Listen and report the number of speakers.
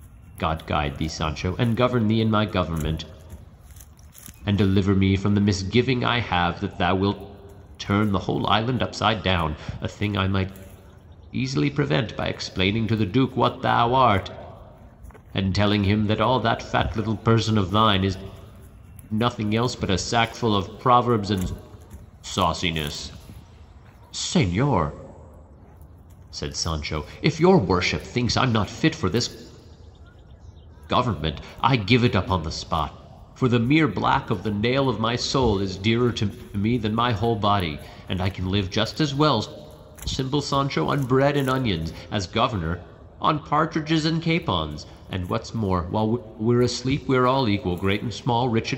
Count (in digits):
1